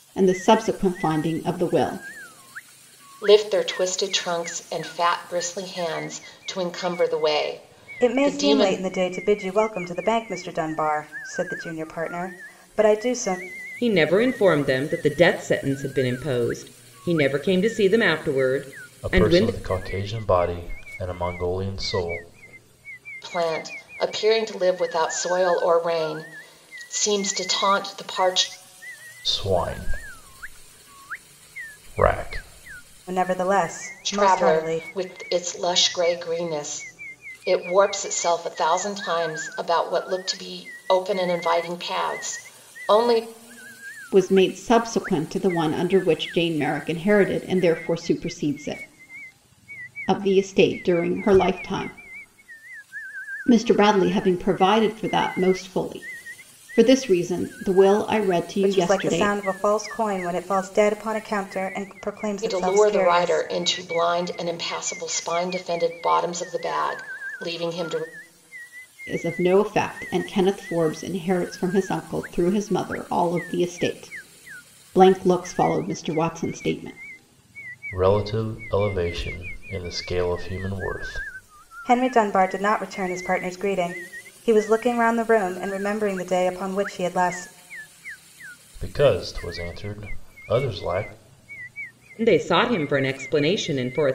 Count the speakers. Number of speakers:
five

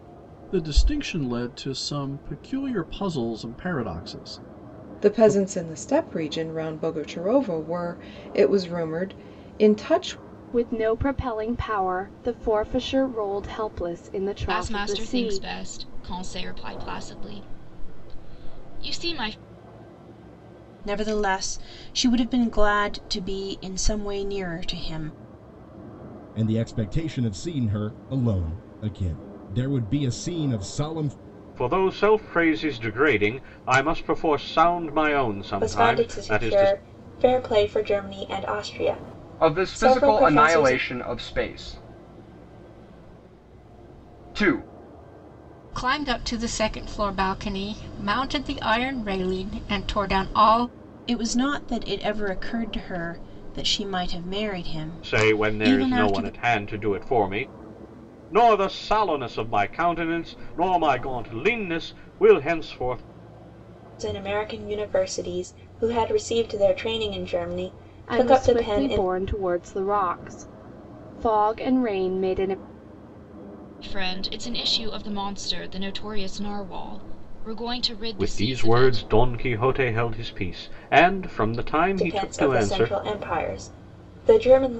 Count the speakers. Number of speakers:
ten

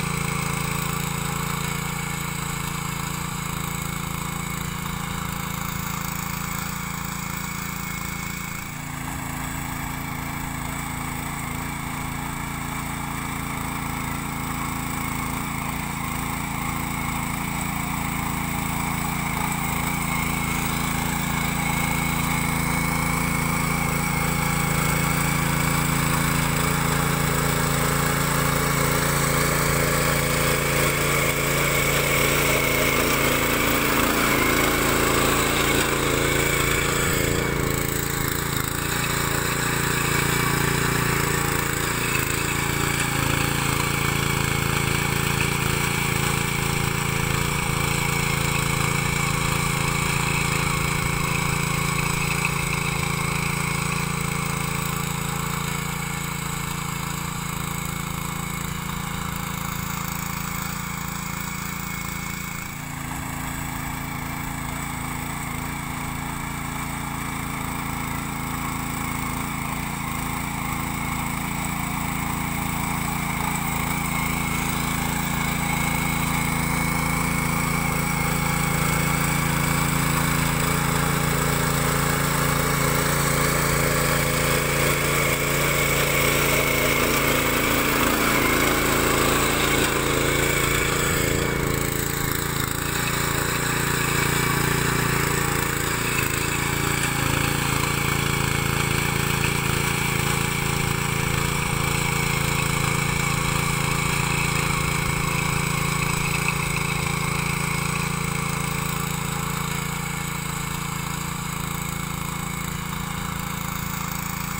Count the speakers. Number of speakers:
zero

